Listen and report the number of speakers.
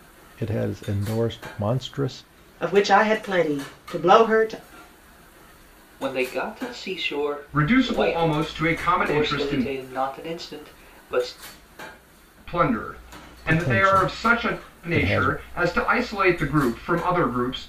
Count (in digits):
4